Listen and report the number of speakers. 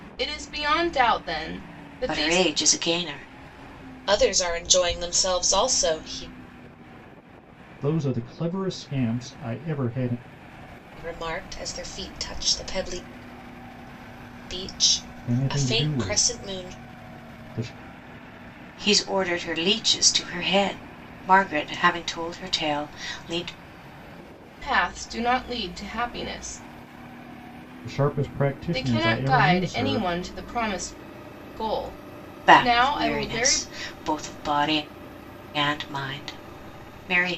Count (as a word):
four